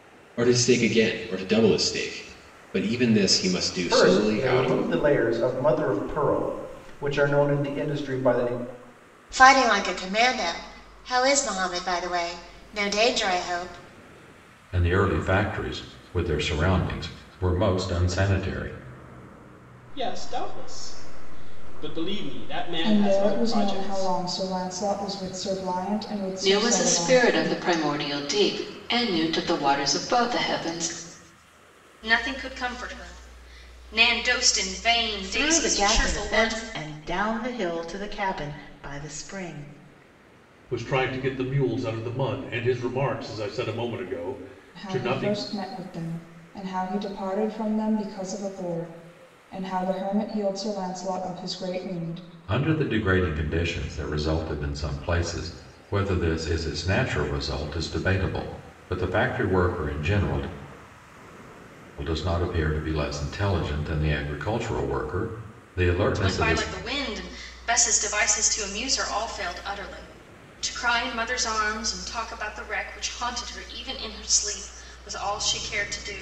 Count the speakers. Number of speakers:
10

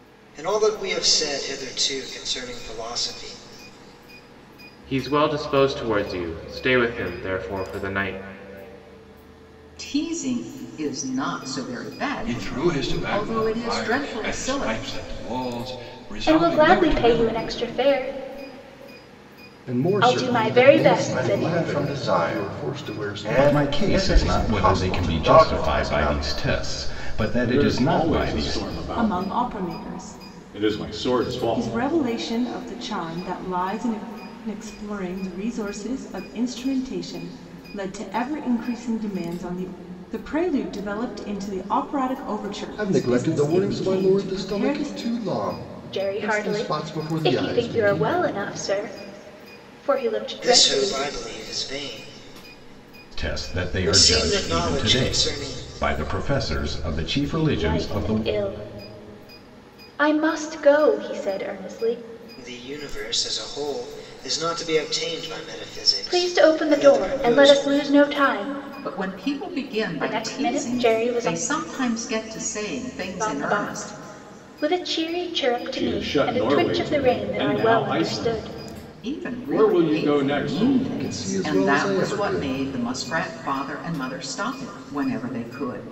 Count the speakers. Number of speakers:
10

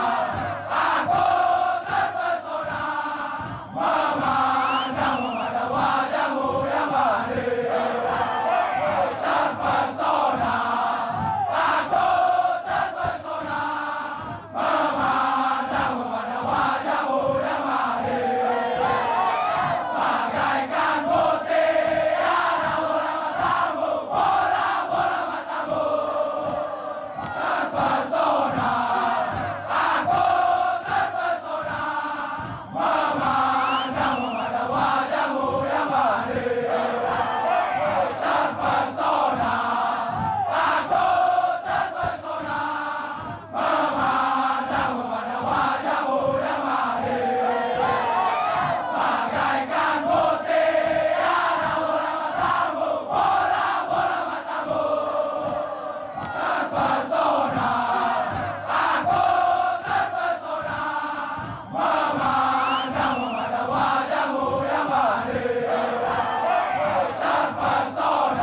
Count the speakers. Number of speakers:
0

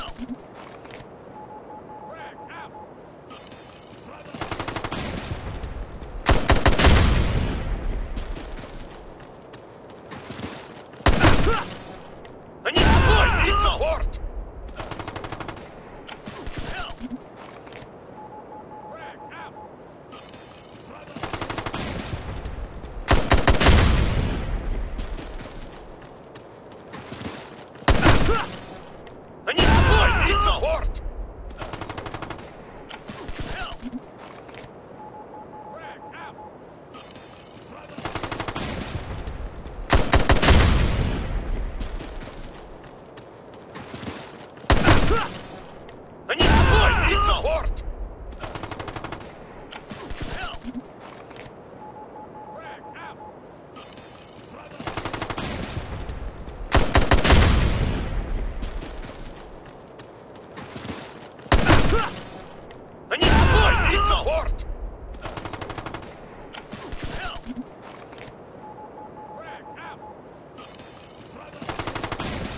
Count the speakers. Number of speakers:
0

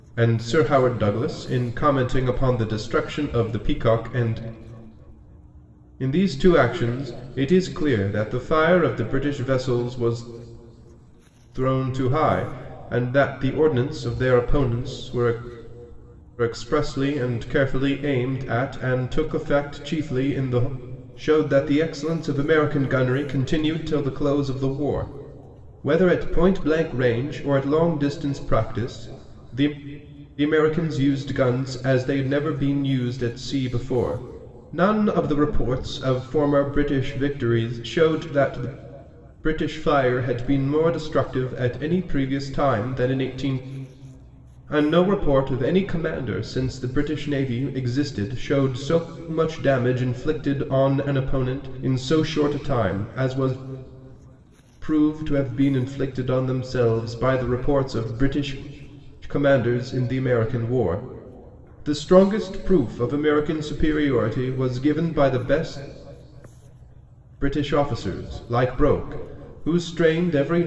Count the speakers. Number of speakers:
1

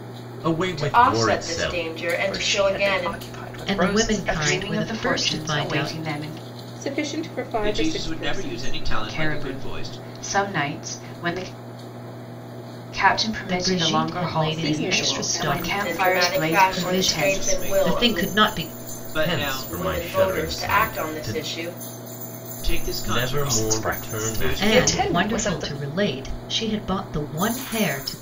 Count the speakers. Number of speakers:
7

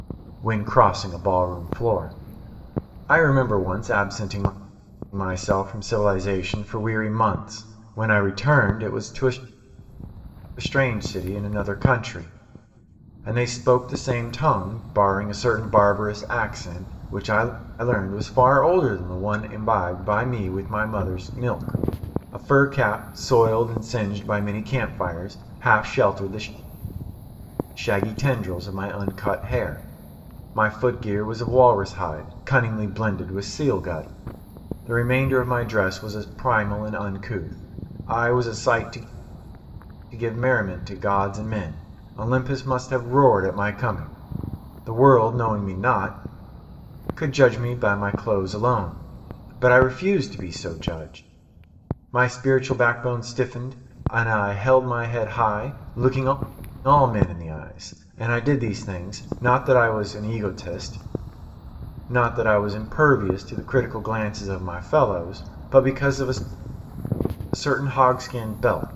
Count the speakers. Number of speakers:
1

